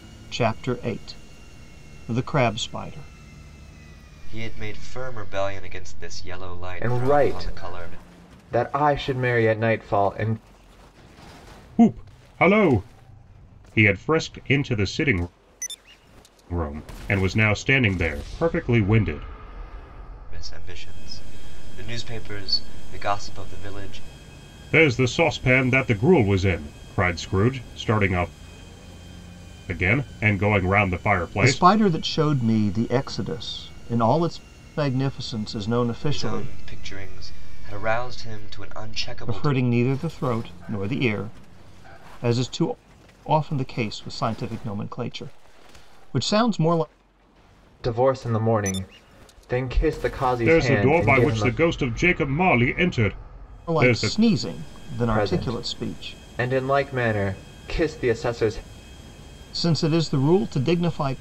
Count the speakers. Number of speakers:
4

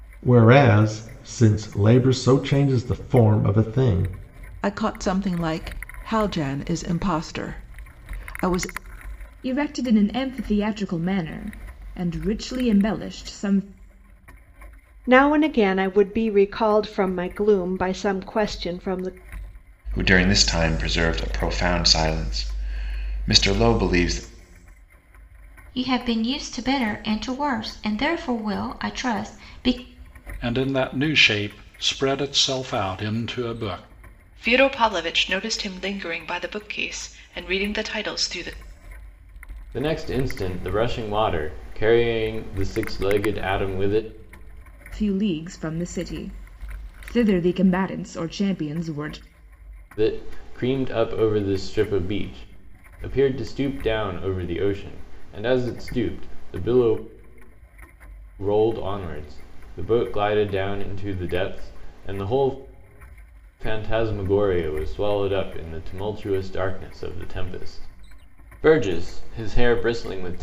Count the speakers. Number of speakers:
9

